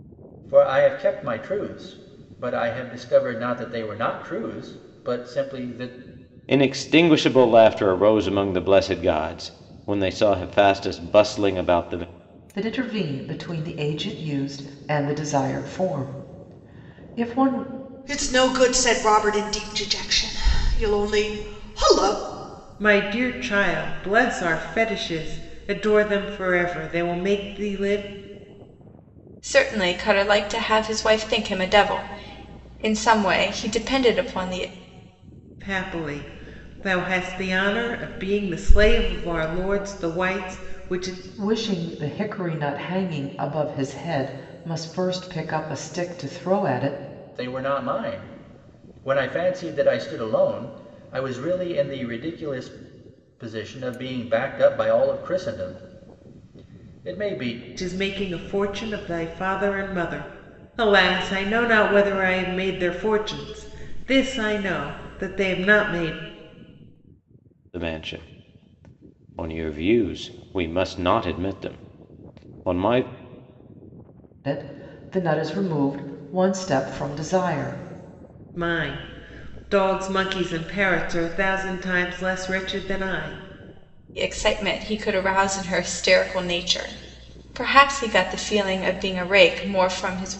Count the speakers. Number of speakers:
6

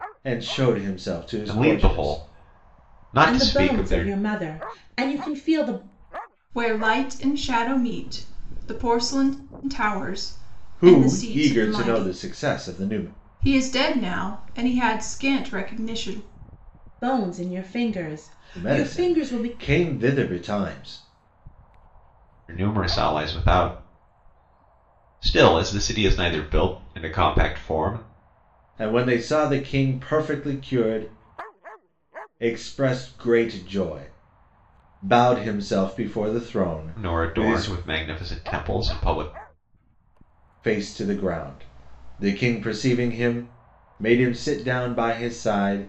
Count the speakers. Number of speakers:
4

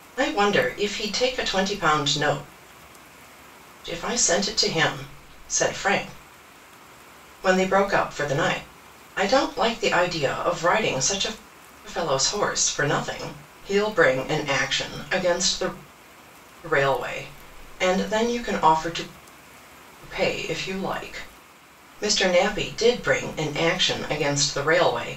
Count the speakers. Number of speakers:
1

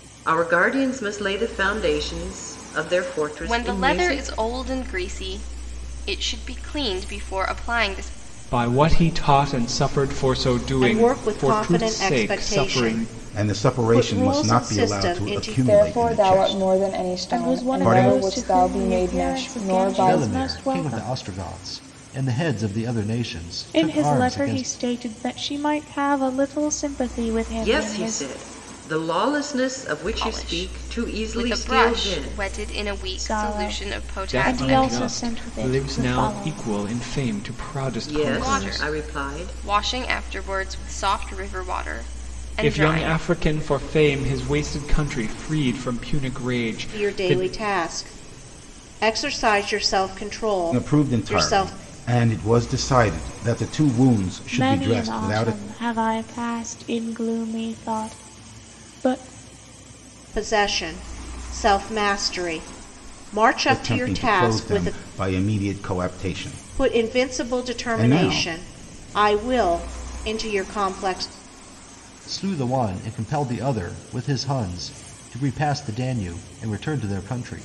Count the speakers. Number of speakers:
8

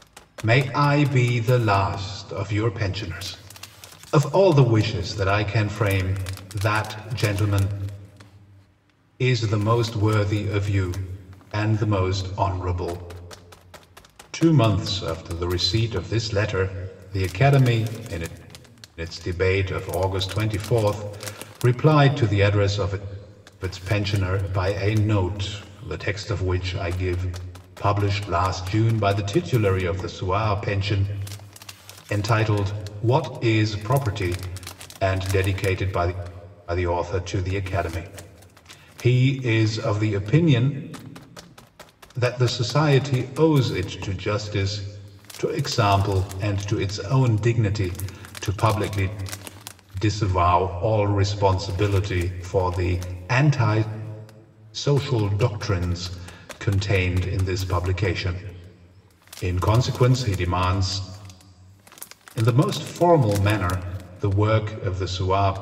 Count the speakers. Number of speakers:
1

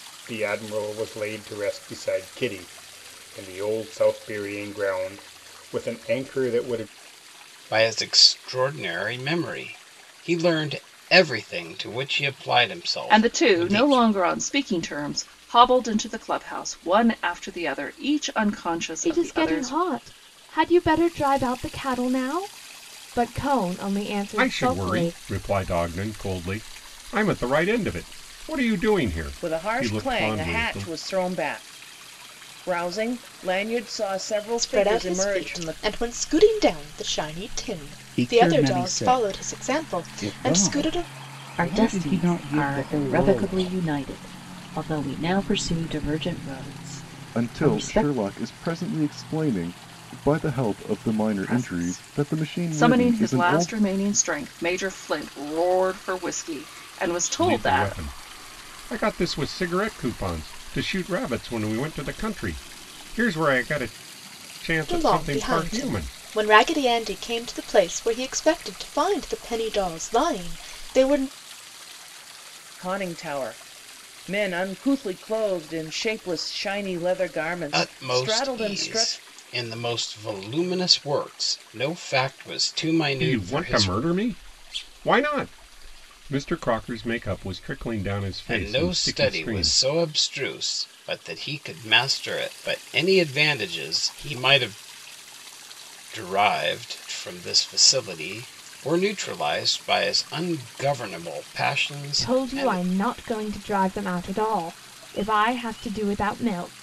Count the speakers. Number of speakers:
10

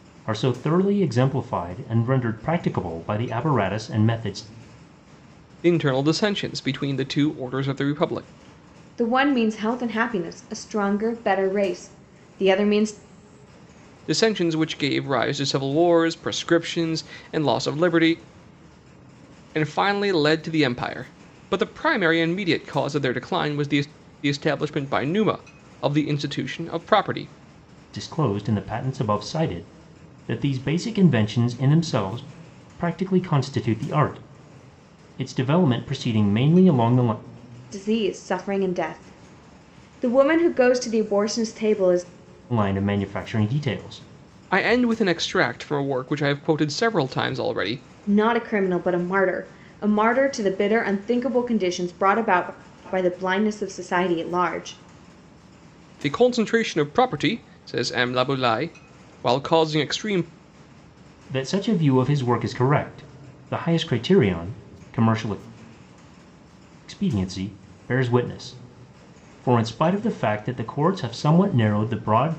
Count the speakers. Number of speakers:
3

